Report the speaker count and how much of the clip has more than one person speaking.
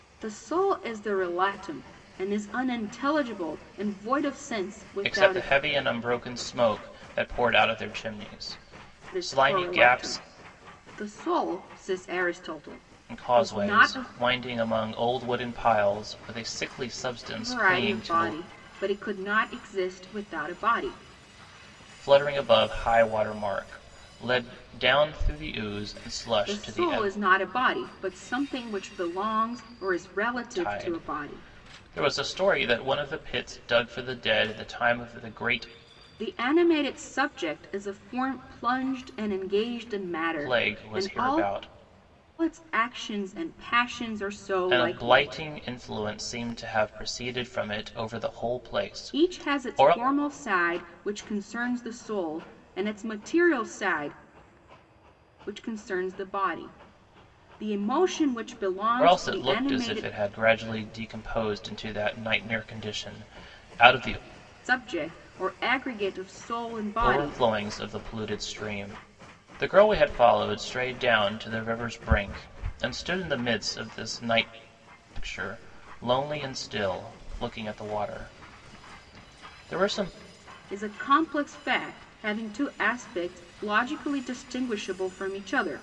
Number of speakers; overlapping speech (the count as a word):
two, about 11%